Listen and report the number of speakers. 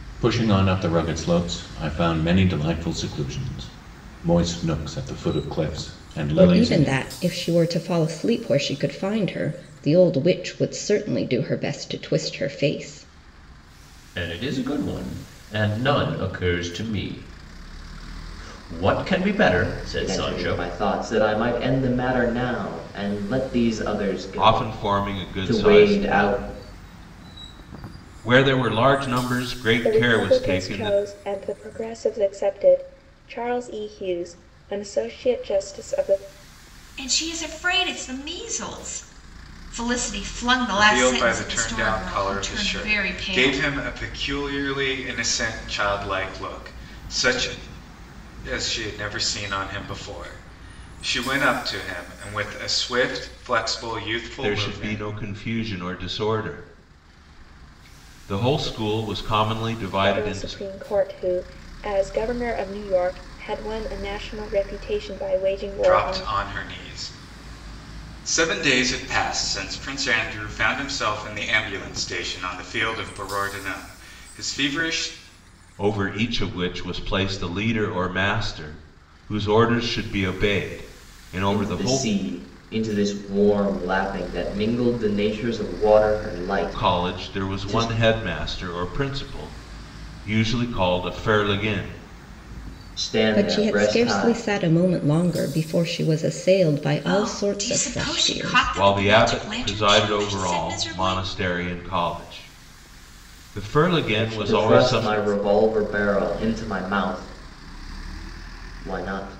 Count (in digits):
8